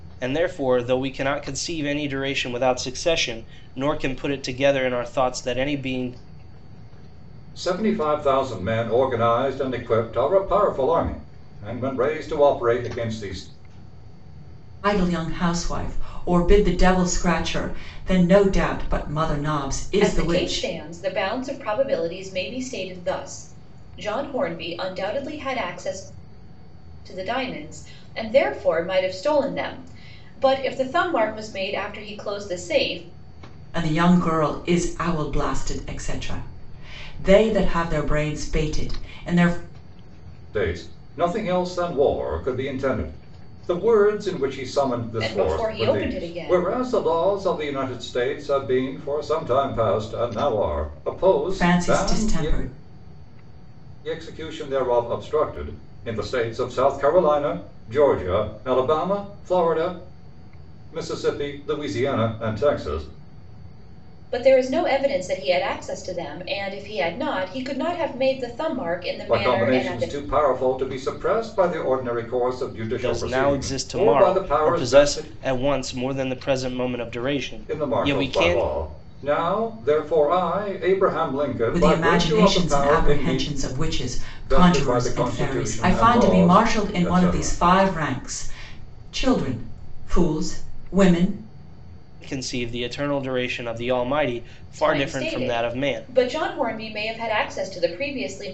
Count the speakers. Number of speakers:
four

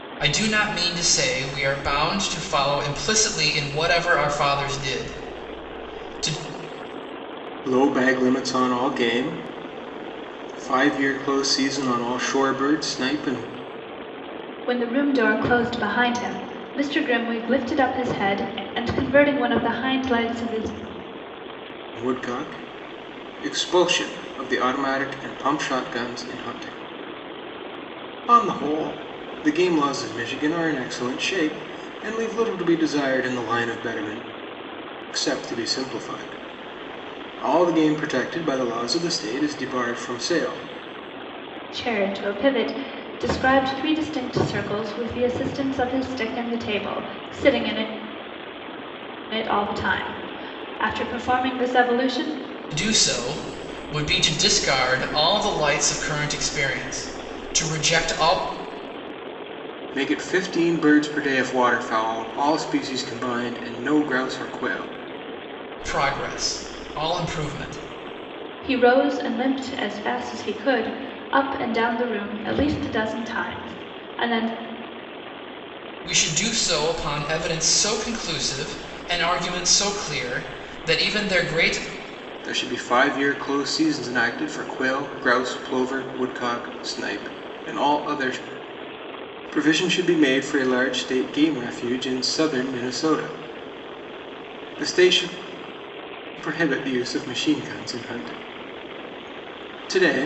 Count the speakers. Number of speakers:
three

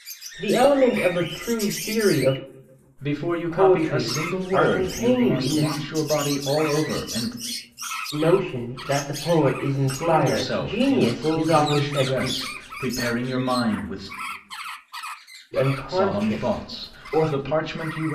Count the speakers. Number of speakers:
two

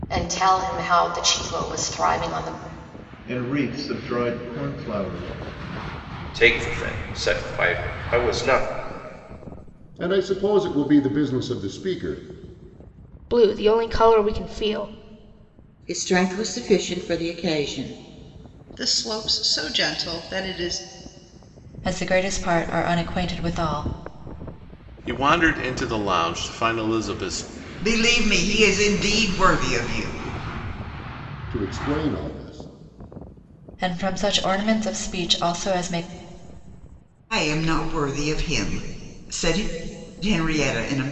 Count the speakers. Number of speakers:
ten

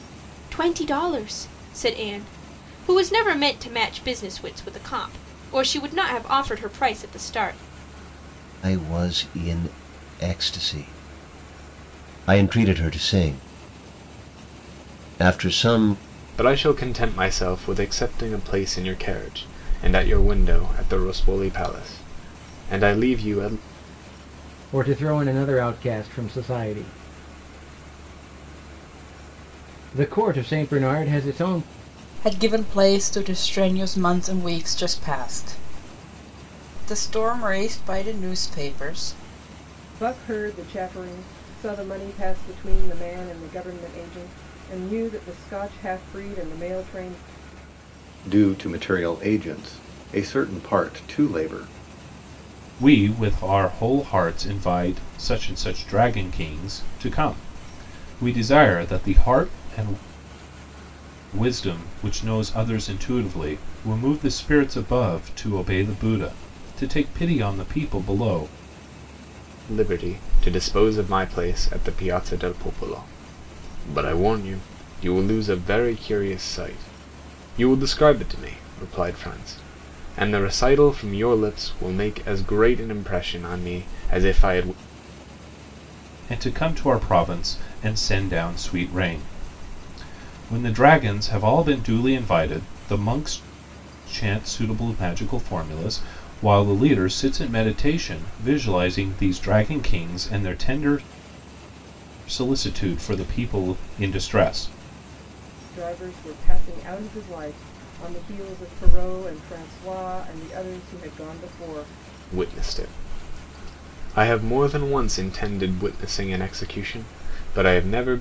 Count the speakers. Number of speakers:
eight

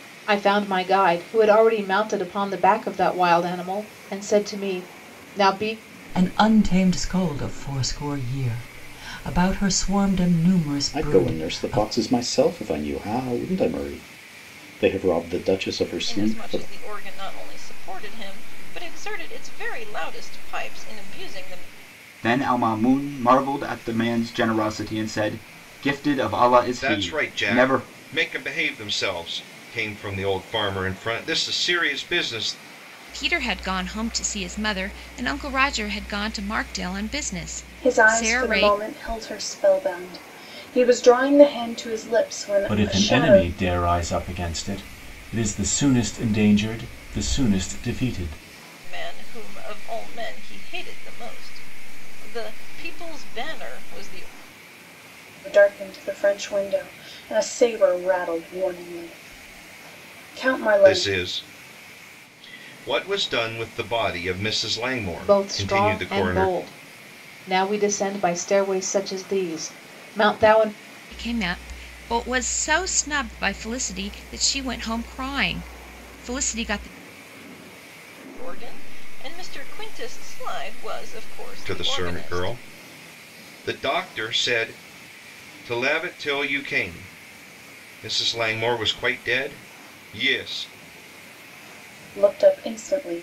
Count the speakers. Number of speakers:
nine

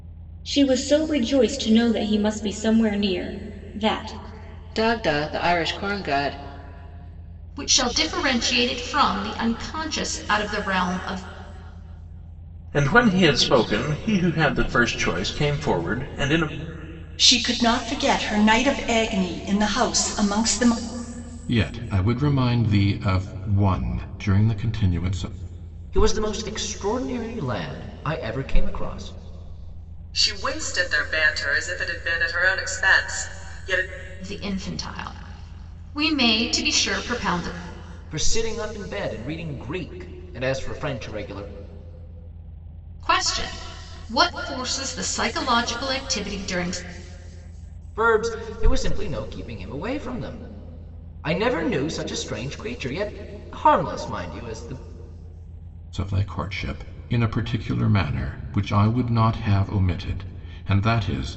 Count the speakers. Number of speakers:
eight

